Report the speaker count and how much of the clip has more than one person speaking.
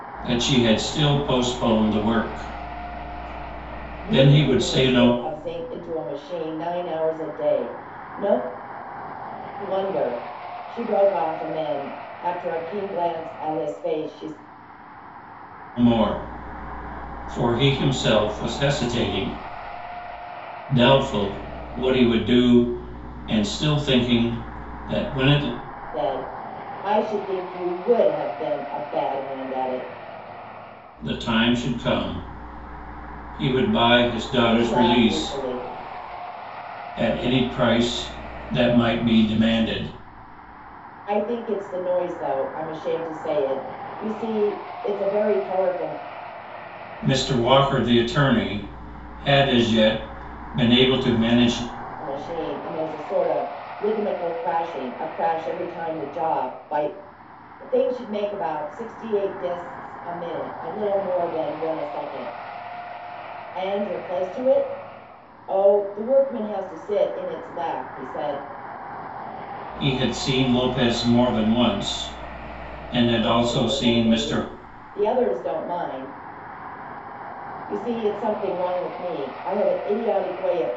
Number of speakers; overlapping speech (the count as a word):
two, about 4%